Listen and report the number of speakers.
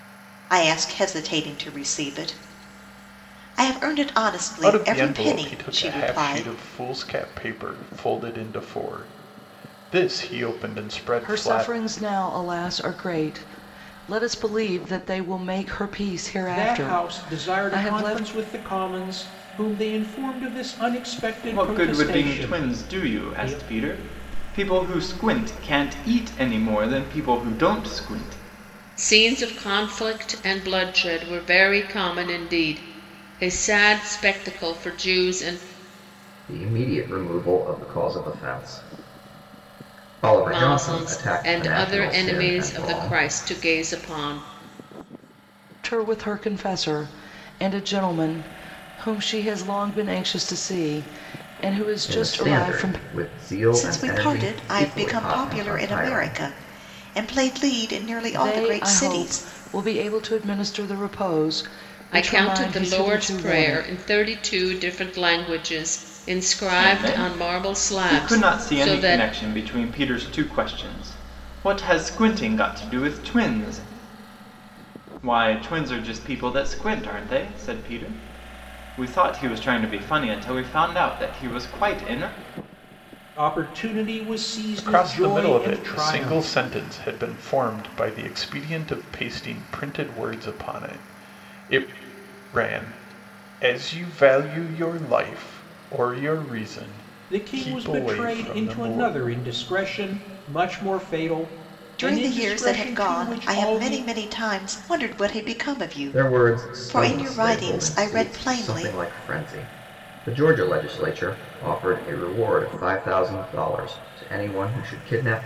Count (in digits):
7